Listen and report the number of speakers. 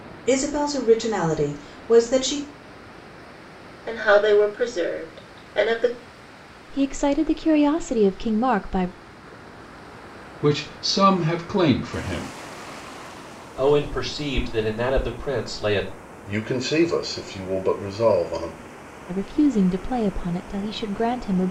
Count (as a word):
six